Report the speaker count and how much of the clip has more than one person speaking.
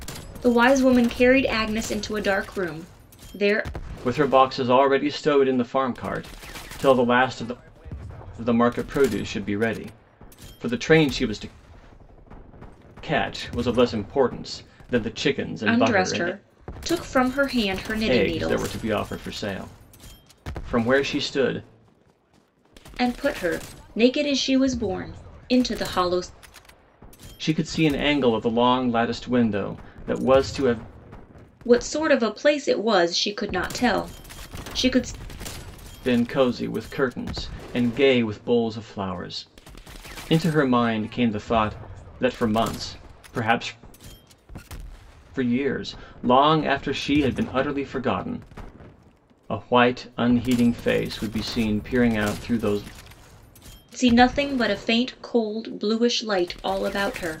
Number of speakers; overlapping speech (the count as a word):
two, about 2%